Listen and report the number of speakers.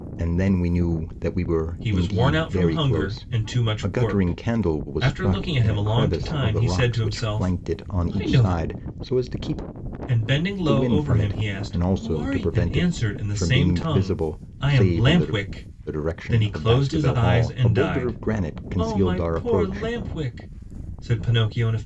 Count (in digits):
2